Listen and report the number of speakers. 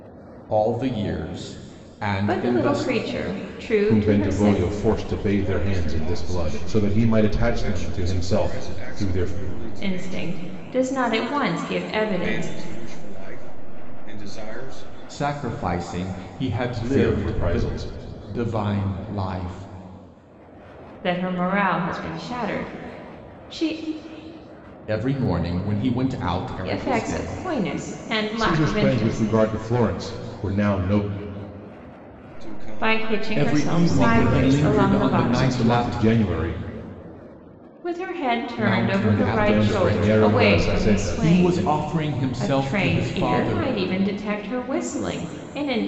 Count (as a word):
four